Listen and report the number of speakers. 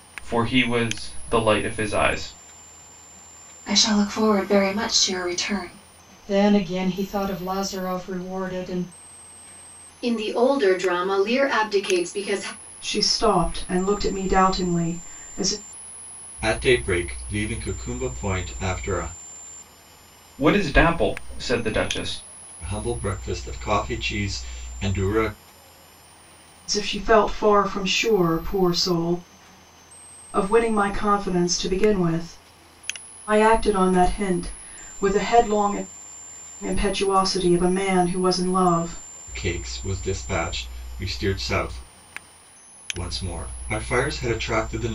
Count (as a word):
six